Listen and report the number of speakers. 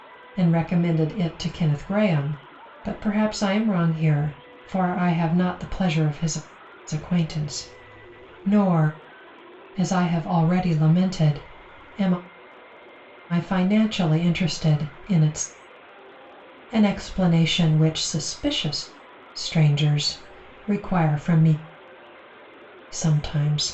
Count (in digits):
1